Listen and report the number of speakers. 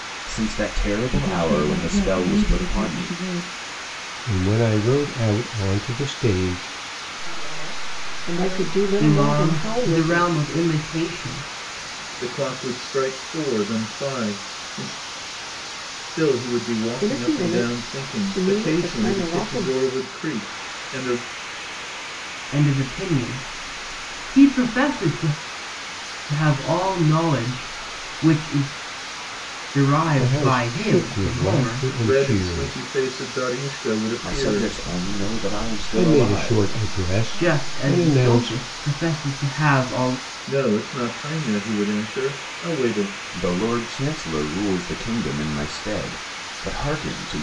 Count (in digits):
7